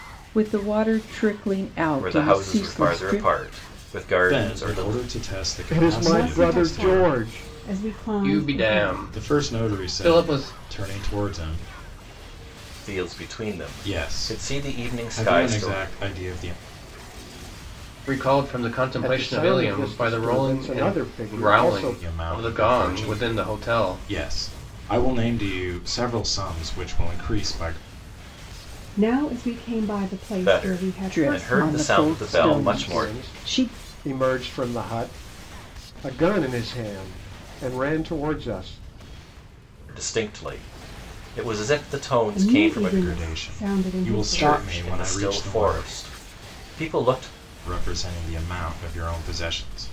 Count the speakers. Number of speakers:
6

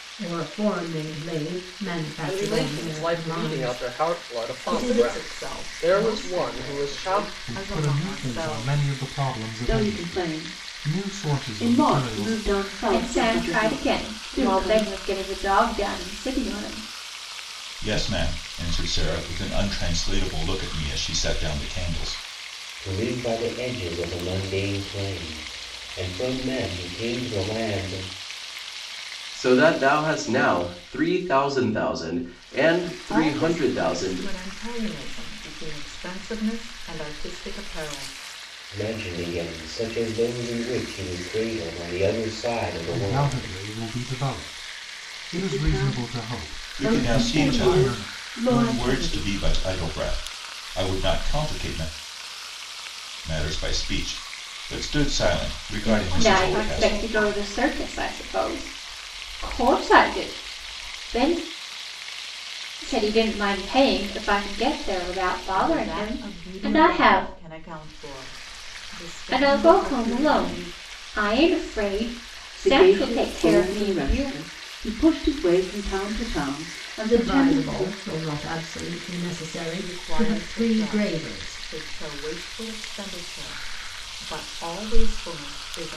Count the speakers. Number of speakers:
9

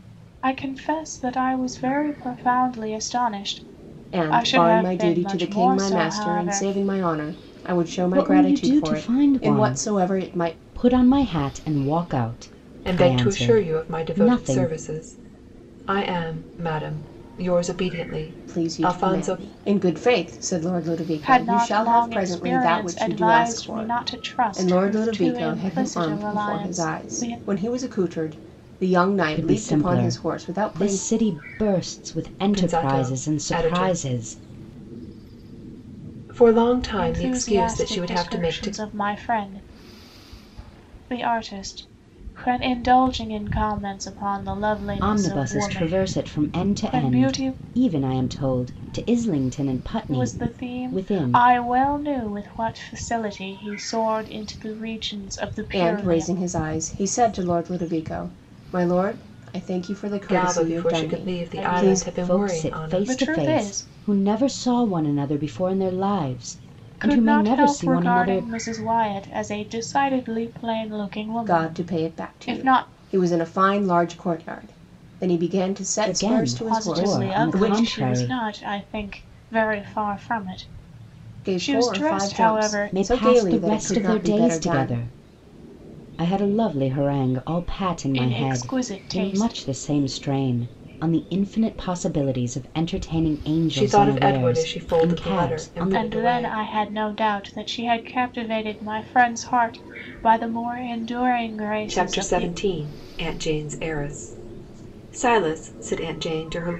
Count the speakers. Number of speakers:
4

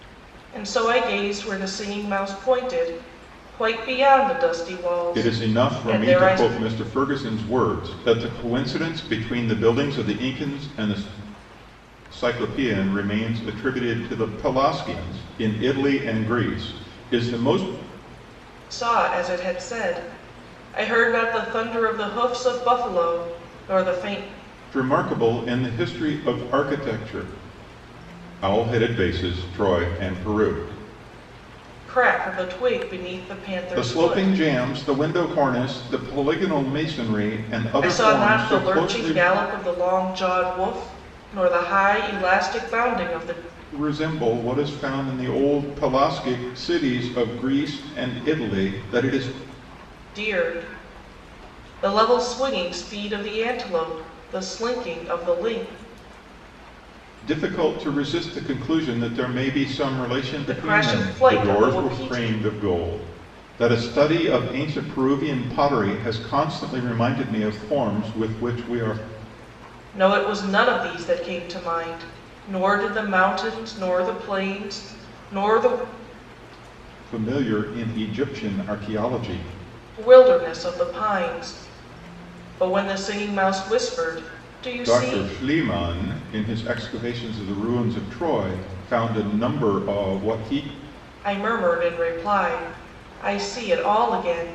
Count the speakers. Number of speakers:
2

